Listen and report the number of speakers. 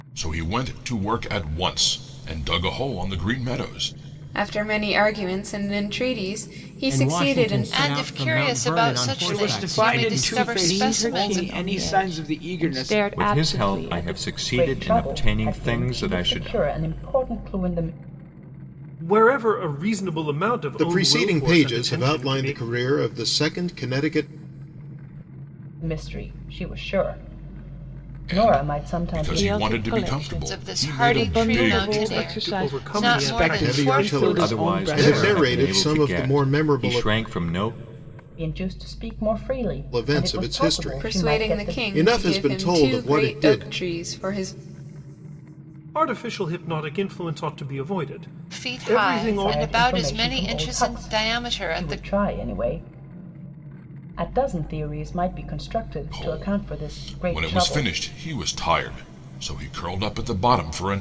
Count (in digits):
10